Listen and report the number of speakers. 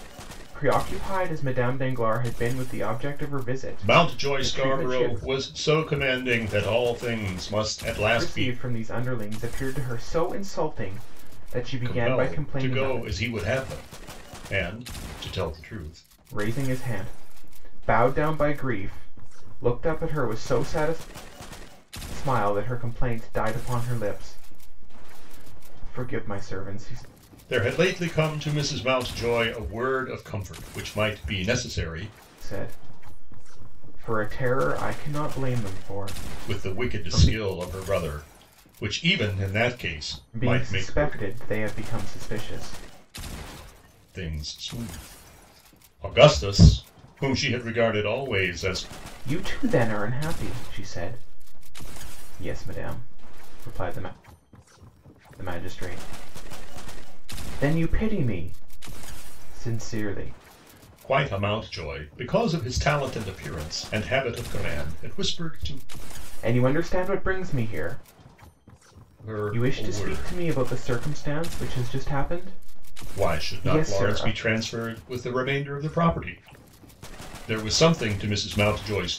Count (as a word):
two